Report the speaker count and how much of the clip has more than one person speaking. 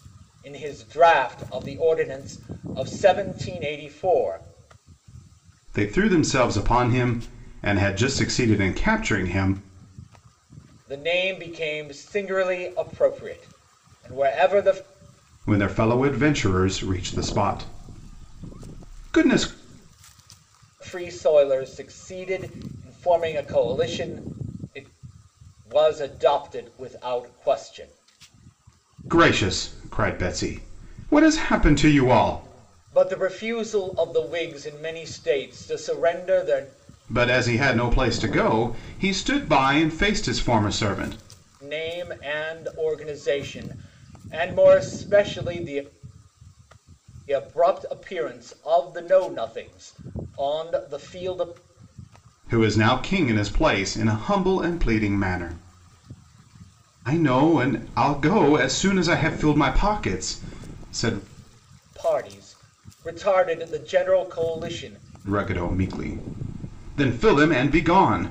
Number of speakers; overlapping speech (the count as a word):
two, no overlap